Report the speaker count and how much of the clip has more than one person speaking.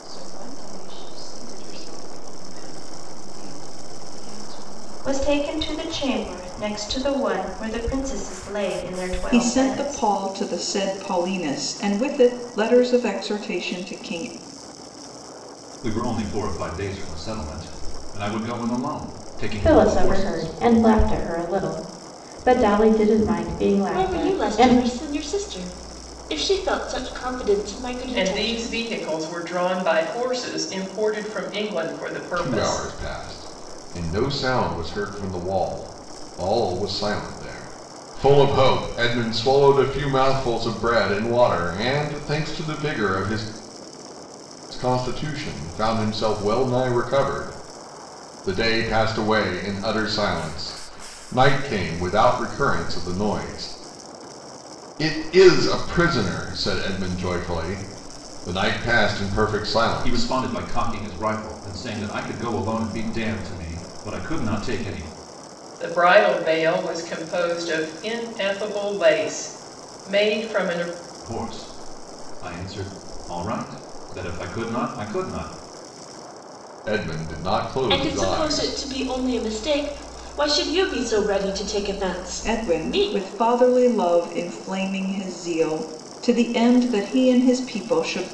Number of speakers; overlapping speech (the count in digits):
8, about 7%